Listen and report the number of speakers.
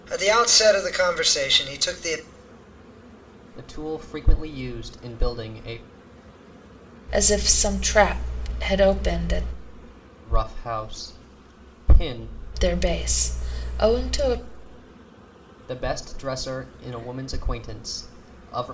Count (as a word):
three